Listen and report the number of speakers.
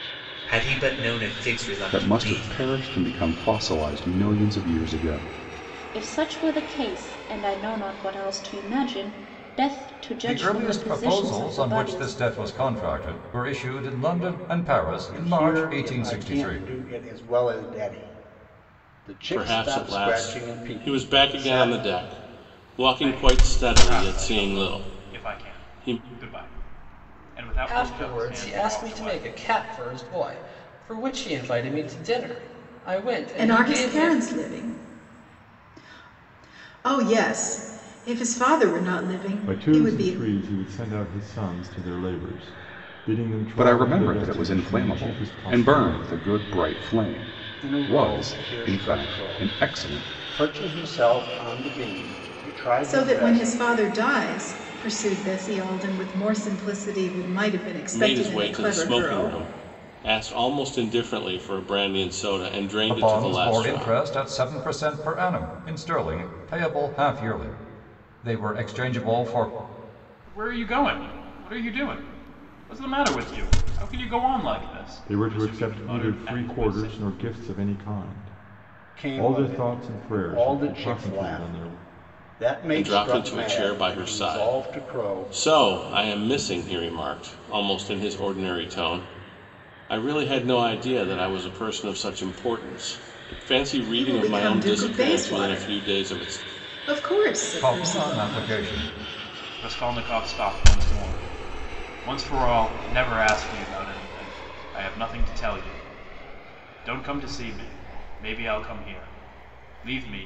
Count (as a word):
ten